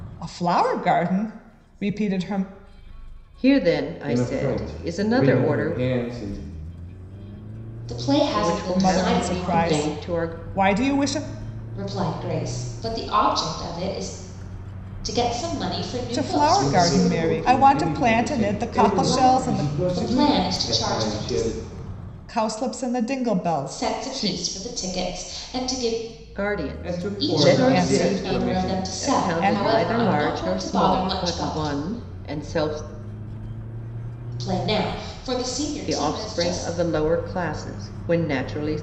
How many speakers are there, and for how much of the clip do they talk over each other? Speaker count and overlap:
four, about 39%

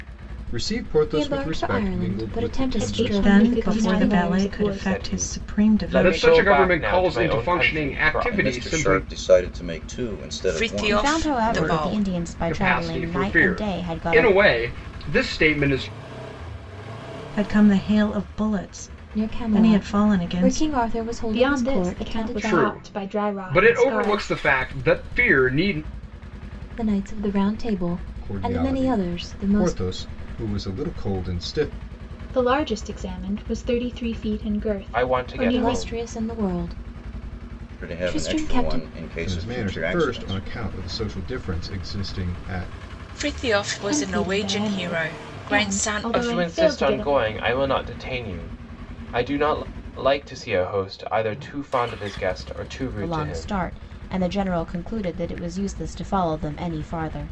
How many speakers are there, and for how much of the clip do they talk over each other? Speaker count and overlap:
nine, about 44%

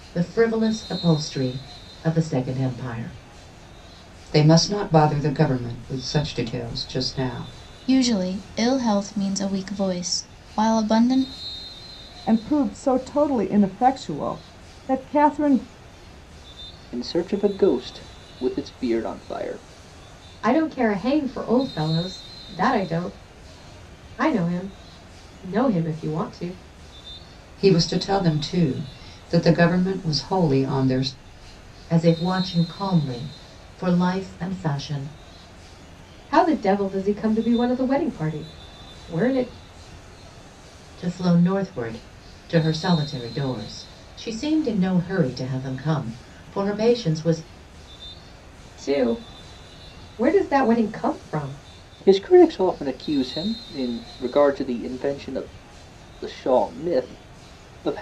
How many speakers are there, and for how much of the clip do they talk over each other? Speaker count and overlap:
six, no overlap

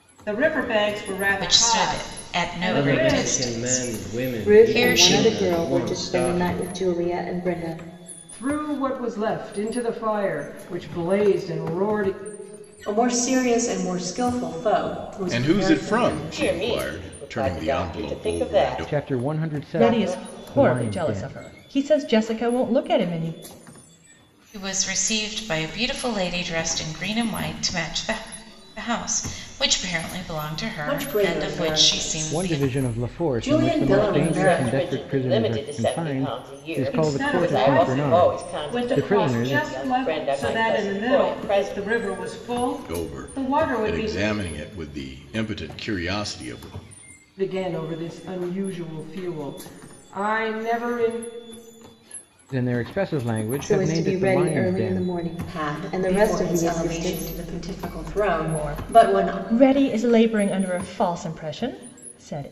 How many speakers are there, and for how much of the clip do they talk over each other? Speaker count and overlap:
ten, about 45%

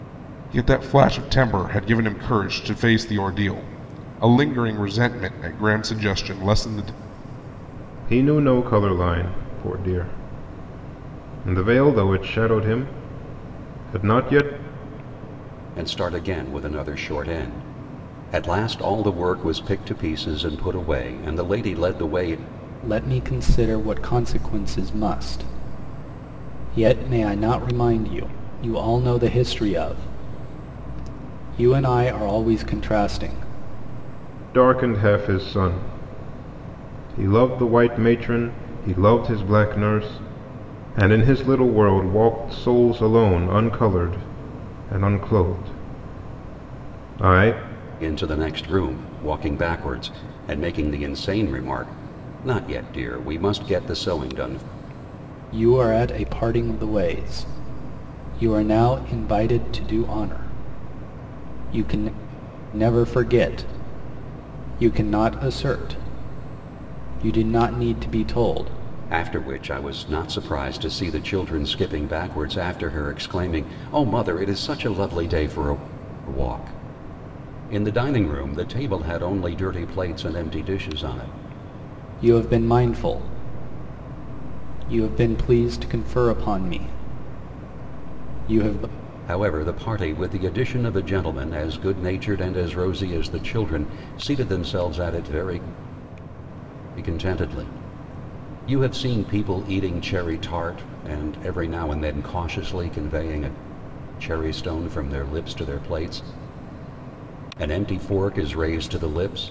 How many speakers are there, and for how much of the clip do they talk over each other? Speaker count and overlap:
four, no overlap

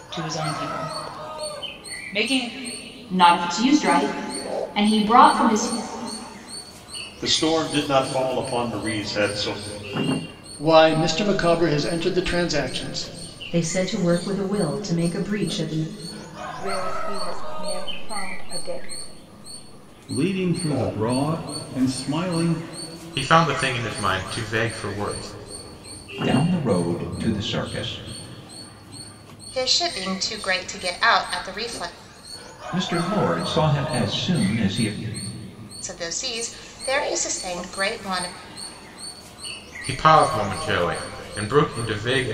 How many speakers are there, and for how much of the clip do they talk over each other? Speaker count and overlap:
ten, no overlap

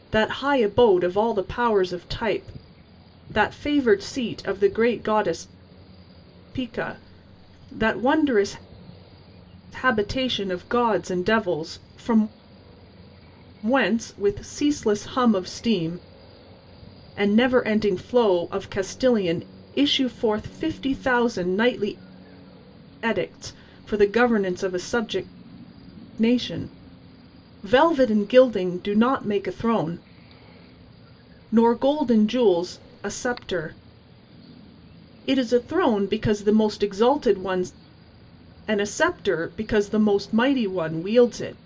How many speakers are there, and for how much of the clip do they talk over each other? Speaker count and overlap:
one, no overlap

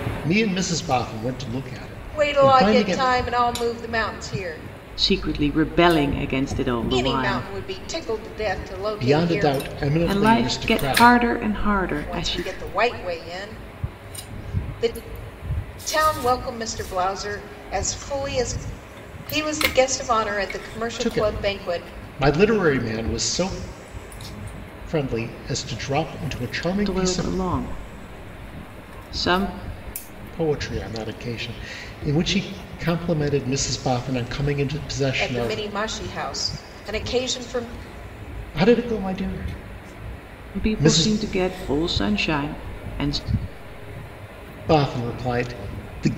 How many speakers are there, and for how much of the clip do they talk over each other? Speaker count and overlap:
three, about 14%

